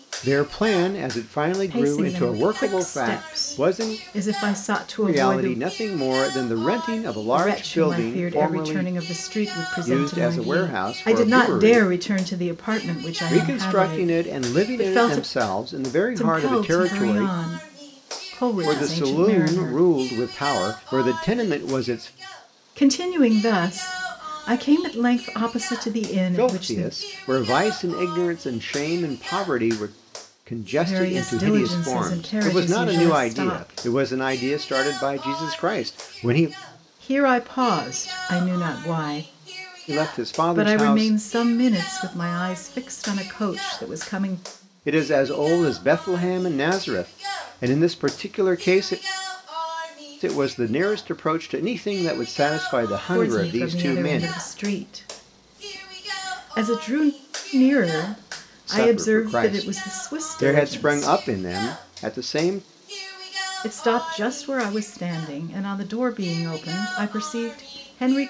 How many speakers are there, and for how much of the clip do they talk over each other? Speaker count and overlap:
two, about 28%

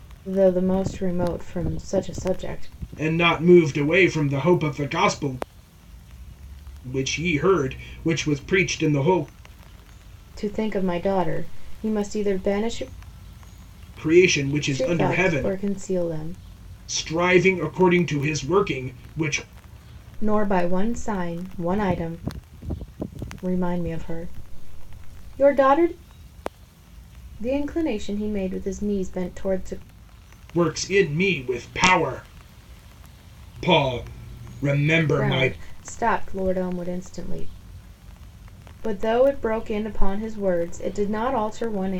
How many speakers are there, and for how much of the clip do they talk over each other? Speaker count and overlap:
two, about 3%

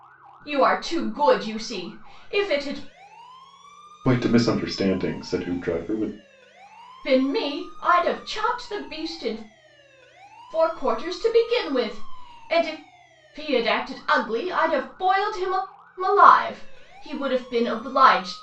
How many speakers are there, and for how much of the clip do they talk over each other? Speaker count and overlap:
two, no overlap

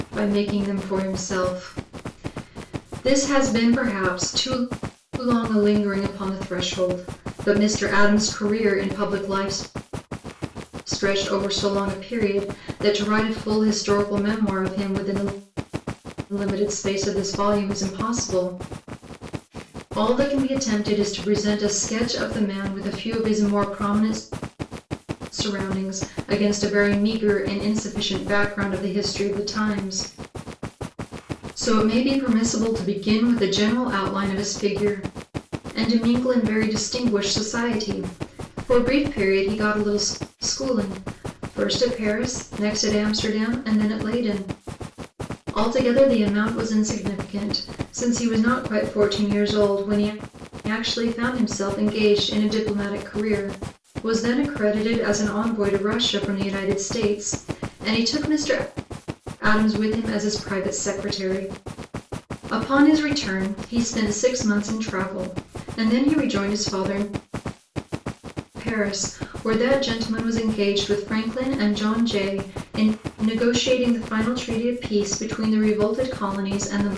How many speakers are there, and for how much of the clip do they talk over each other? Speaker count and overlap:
one, no overlap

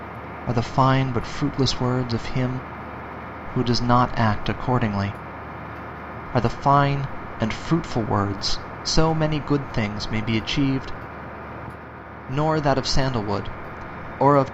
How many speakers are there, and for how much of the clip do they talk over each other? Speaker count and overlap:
one, no overlap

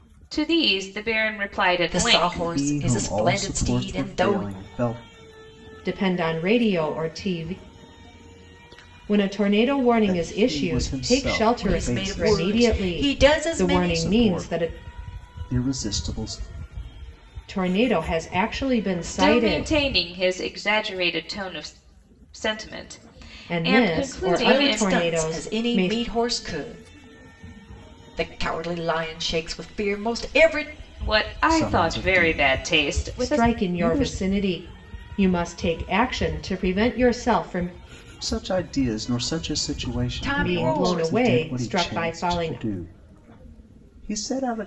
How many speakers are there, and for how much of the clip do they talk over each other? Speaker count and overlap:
four, about 35%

